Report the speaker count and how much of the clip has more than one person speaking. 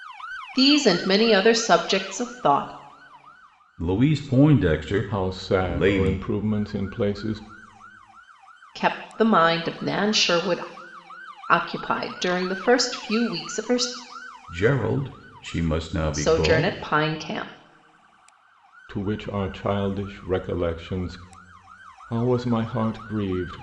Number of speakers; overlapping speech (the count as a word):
three, about 8%